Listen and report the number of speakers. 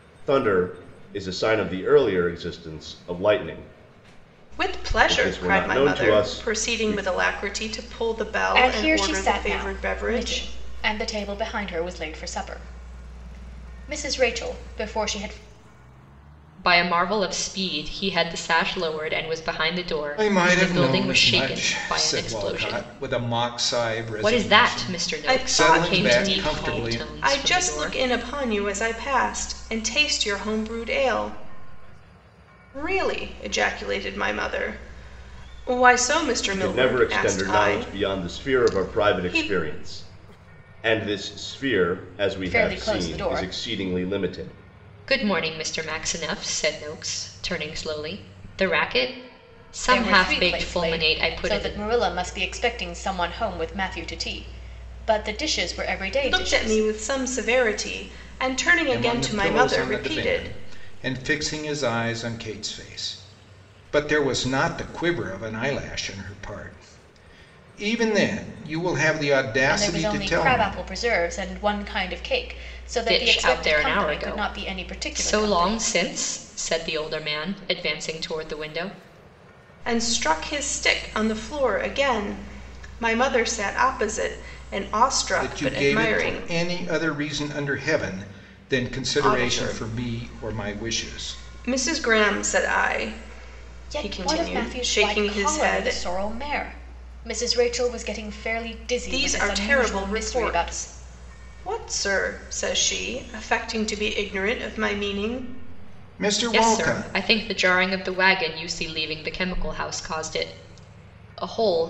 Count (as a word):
five